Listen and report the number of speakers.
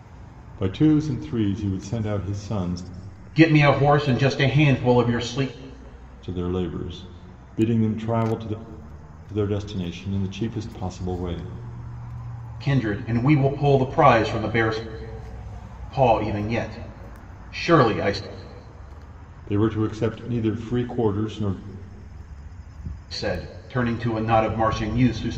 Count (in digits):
2